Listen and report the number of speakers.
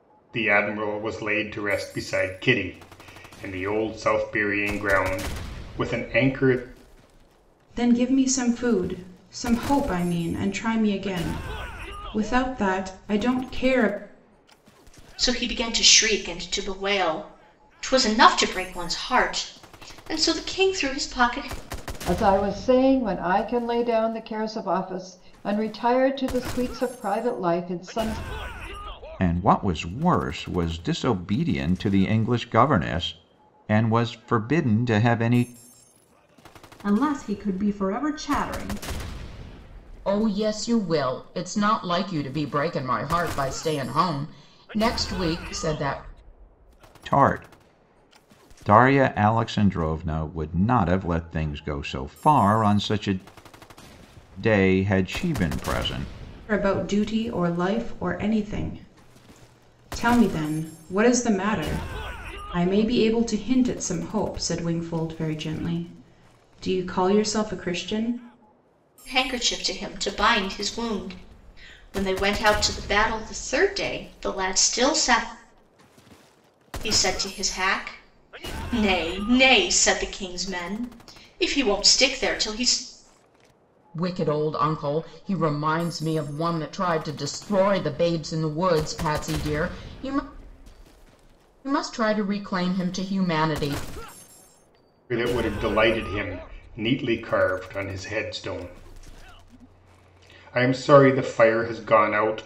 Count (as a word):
seven